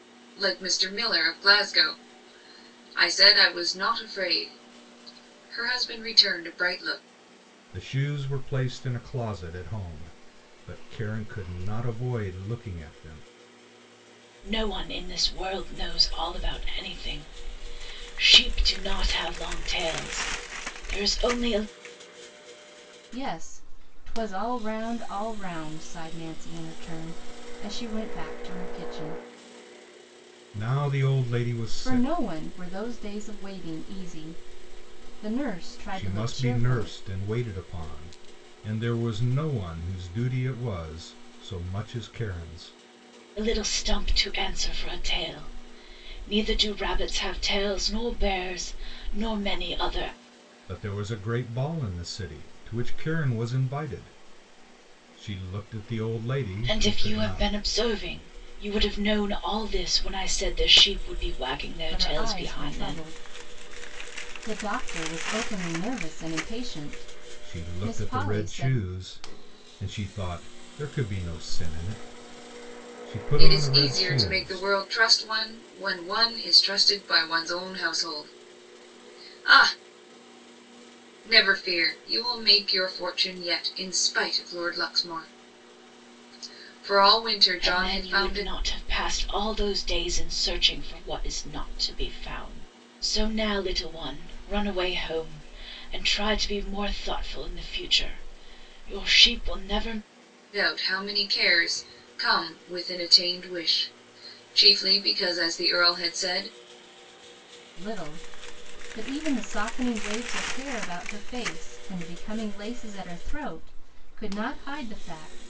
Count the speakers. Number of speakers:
four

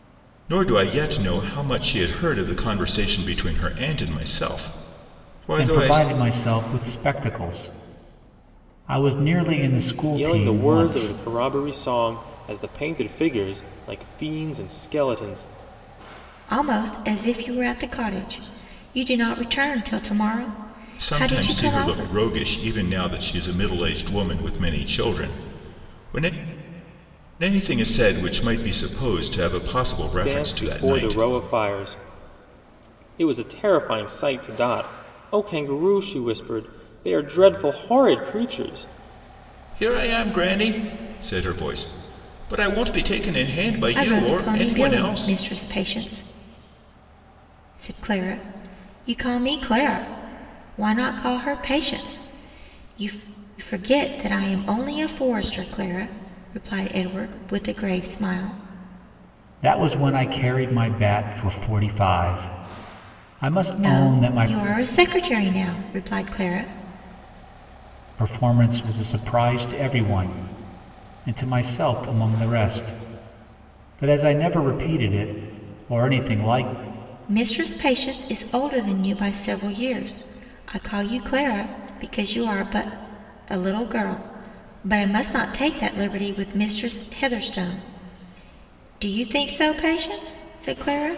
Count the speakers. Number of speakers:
four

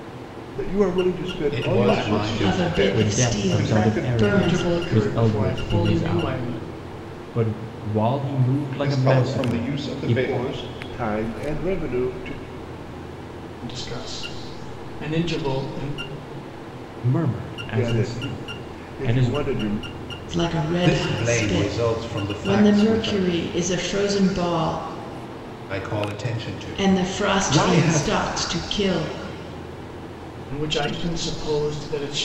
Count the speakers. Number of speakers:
six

